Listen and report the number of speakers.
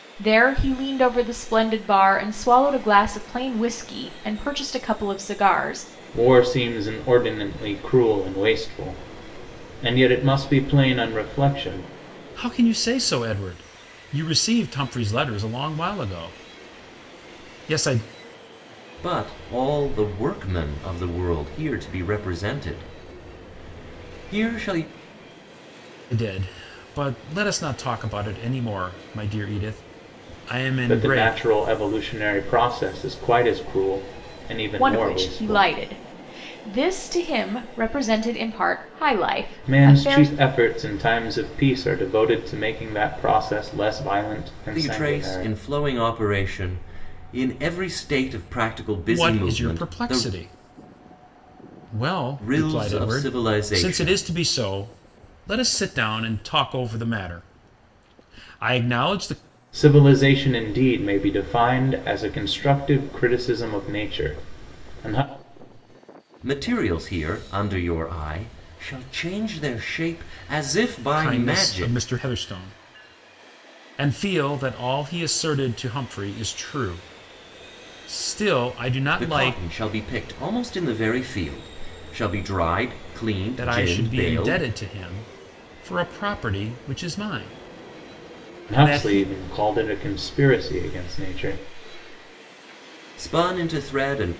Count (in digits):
4